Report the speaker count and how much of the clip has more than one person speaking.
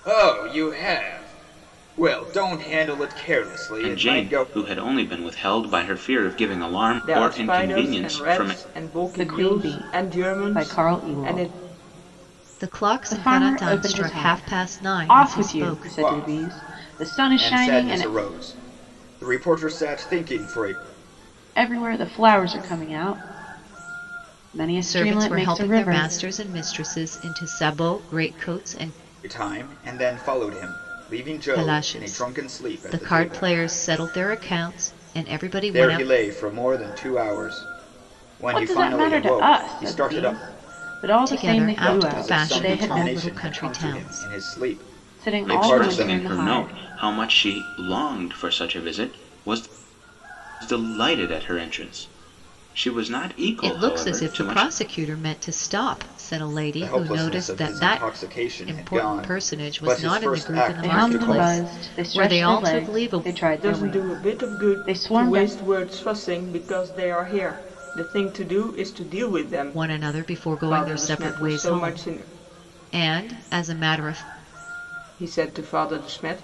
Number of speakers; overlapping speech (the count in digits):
5, about 42%